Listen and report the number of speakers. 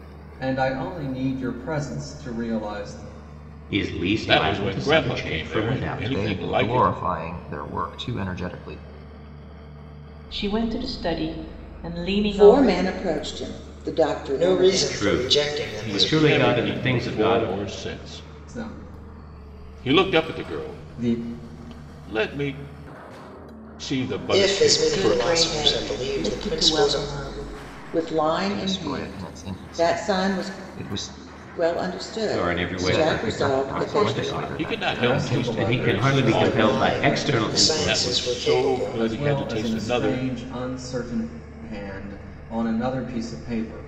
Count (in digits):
7